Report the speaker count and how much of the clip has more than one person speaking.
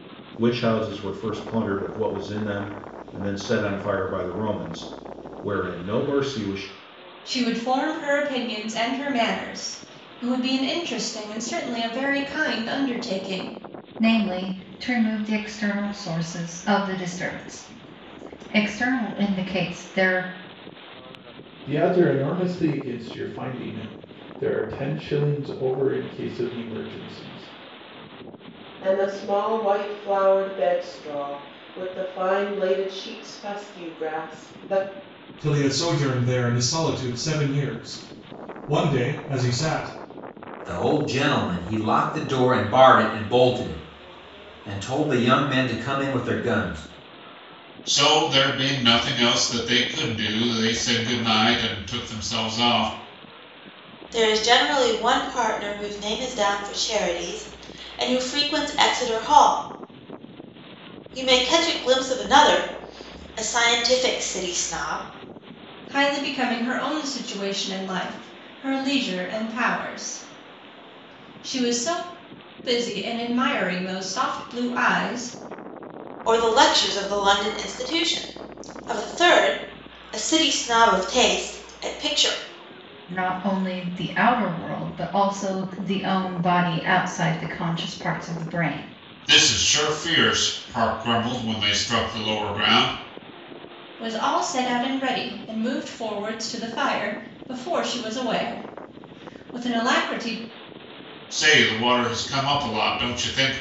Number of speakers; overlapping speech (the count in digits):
9, no overlap